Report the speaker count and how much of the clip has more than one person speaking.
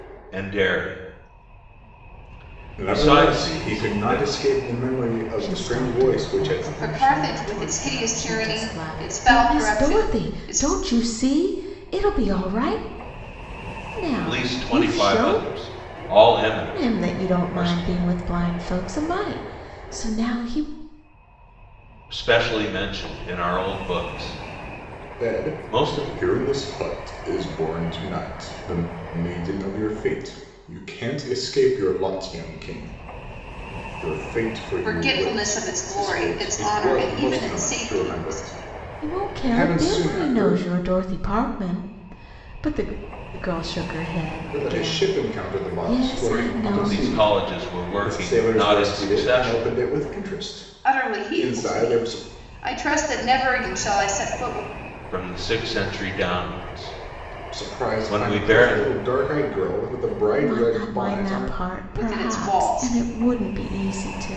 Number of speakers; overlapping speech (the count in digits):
4, about 39%